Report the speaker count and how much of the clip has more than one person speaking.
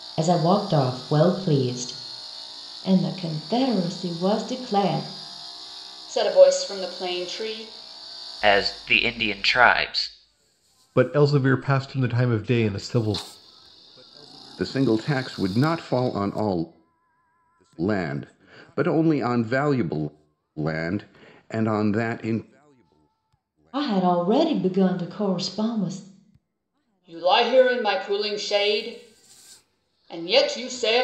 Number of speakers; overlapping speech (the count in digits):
6, no overlap